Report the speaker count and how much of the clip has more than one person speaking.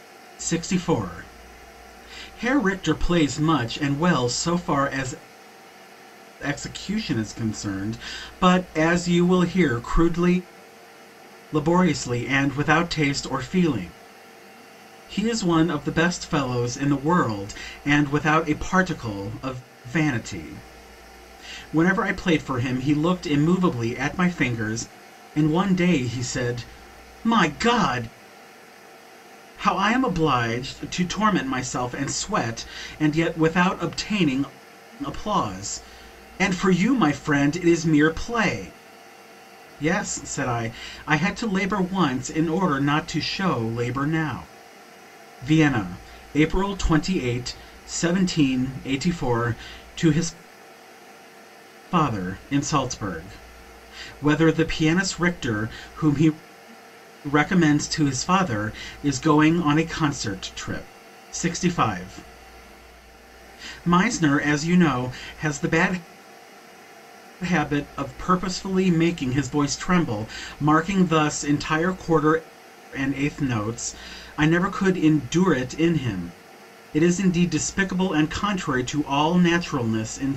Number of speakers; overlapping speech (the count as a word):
one, no overlap